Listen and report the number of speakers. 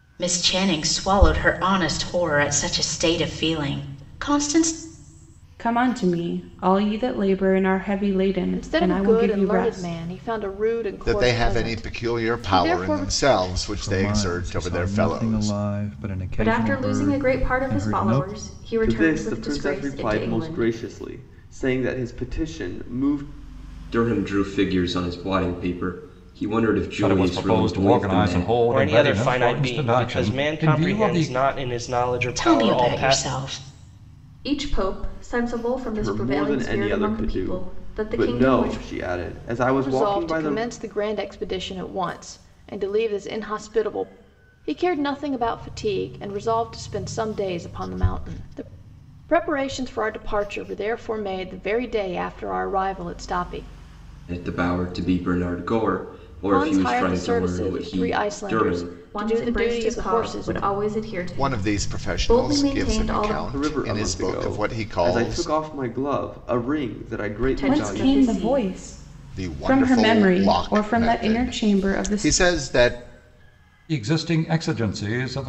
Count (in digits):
10